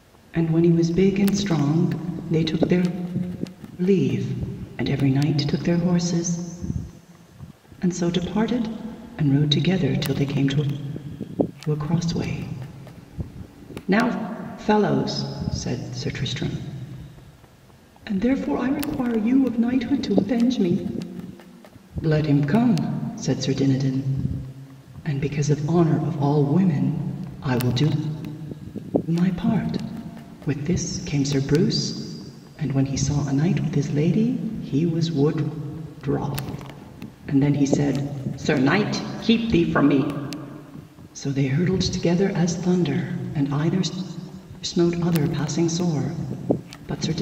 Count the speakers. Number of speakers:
one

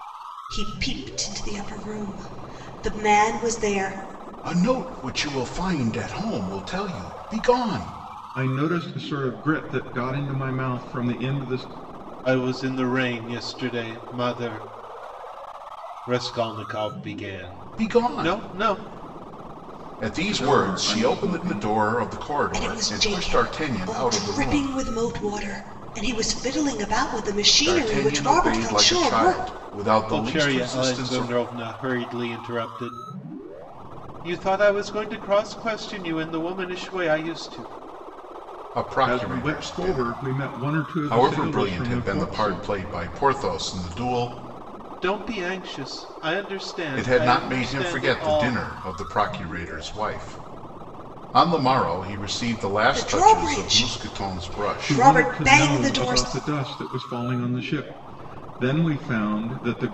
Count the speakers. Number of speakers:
four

